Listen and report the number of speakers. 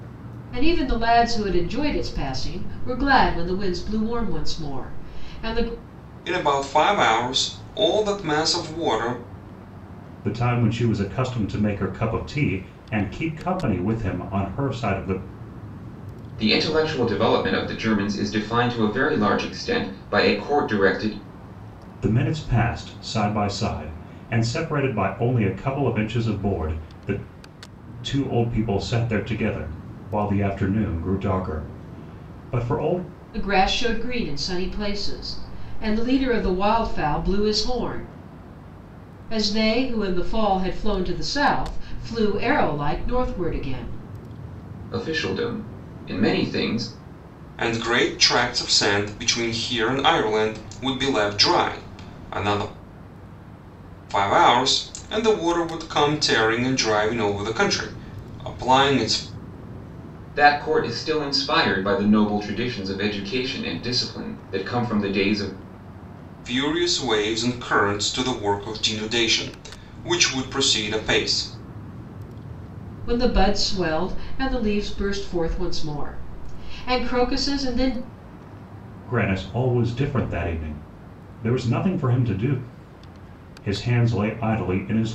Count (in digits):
4